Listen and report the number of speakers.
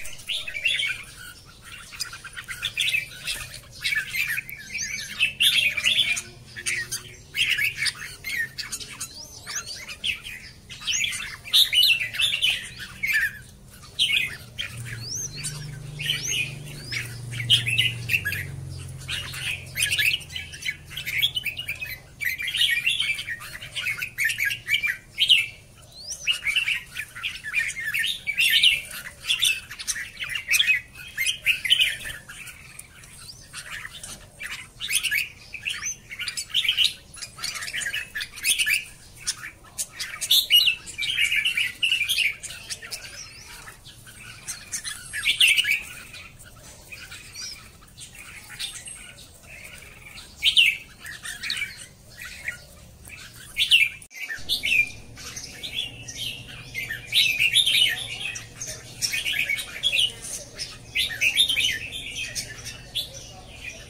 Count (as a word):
zero